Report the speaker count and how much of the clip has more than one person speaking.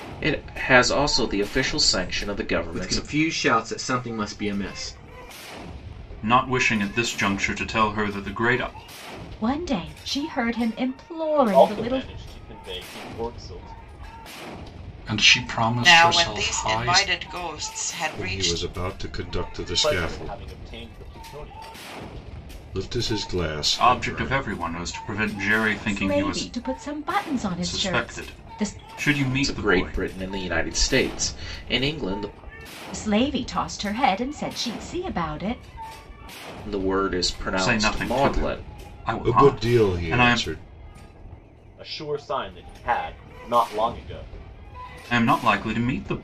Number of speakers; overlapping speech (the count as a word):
eight, about 20%